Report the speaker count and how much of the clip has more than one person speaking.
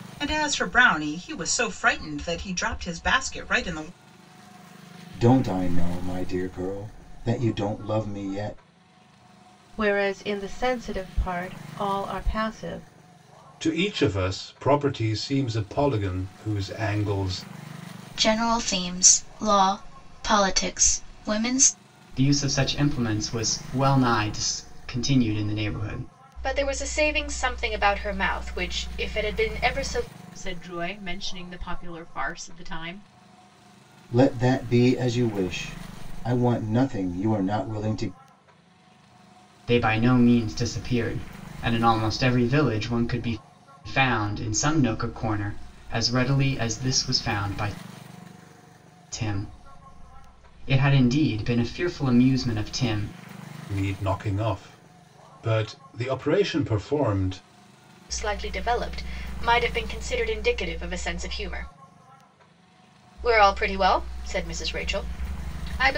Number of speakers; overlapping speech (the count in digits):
8, no overlap